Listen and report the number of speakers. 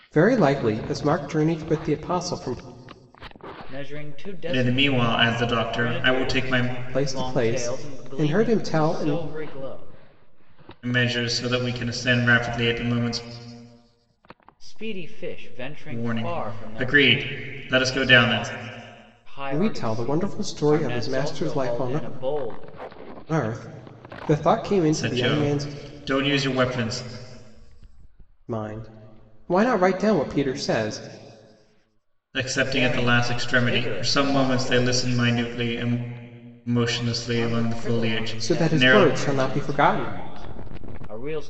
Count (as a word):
three